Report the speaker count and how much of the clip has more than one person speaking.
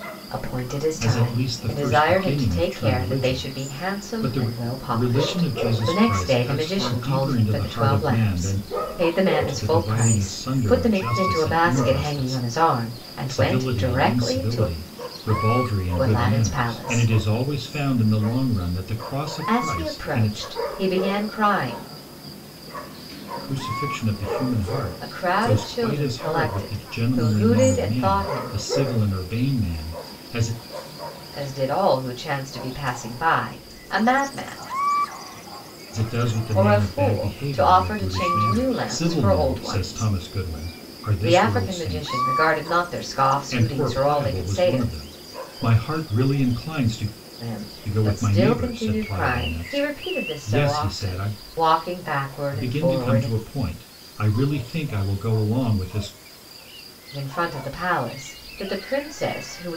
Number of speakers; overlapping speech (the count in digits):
2, about 47%